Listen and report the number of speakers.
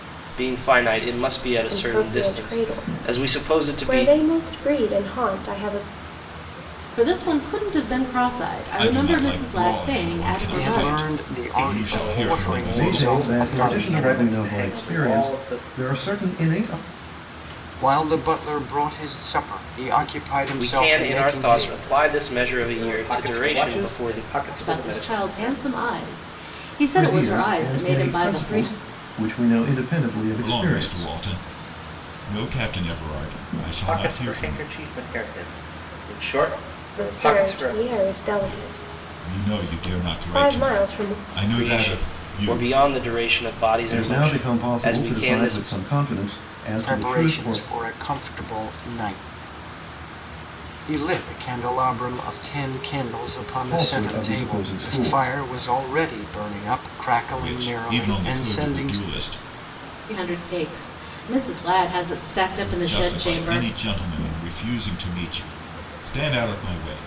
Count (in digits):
7